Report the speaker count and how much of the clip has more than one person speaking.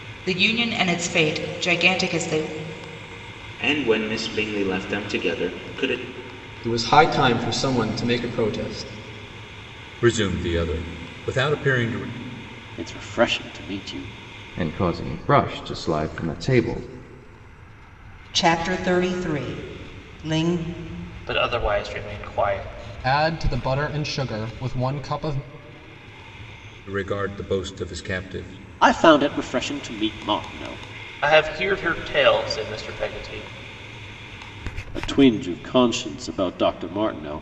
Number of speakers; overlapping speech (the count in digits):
9, no overlap